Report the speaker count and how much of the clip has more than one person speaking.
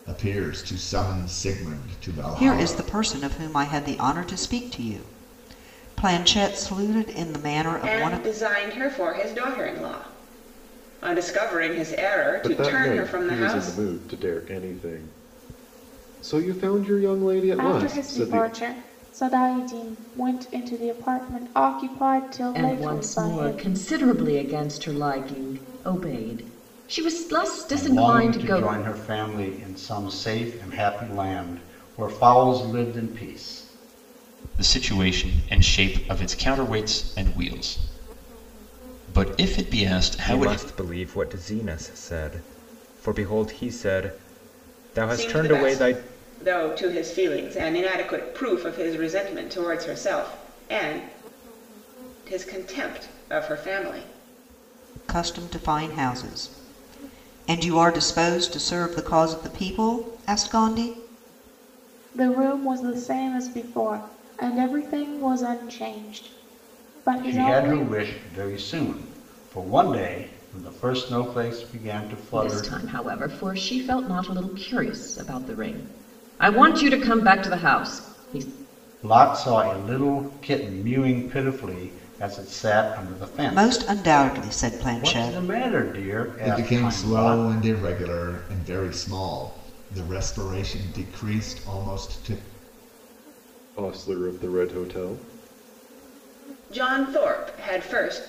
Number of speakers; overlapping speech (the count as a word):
nine, about 10%